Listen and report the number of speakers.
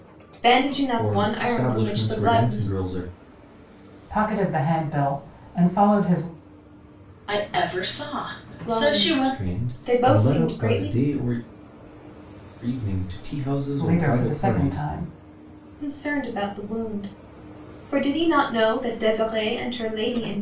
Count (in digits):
4